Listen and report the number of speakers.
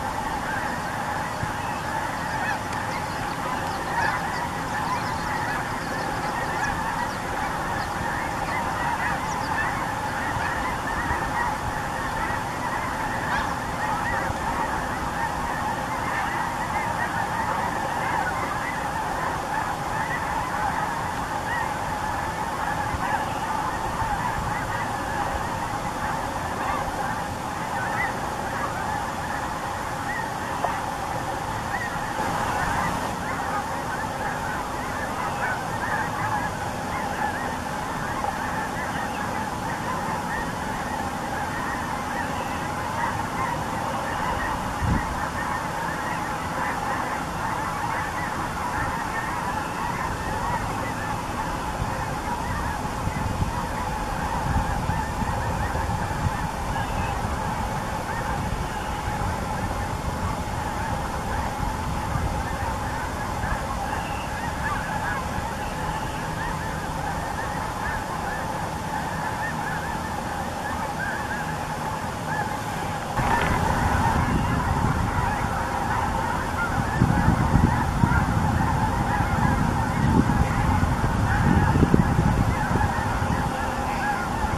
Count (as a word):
zero